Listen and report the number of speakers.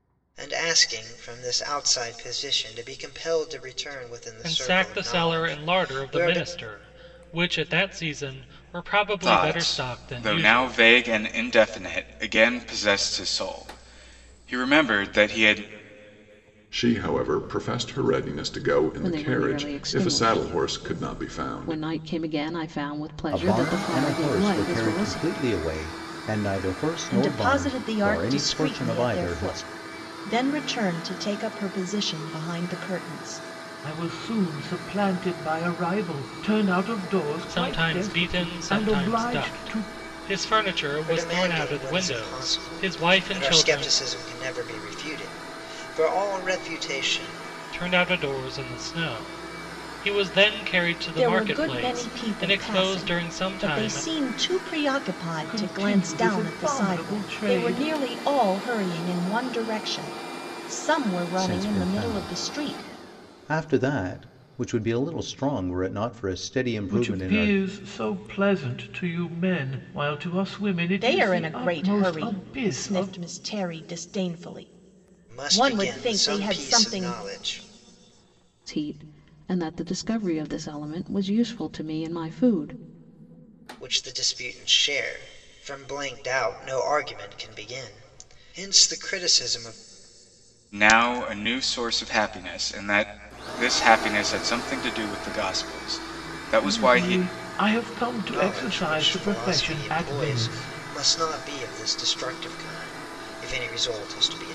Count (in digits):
8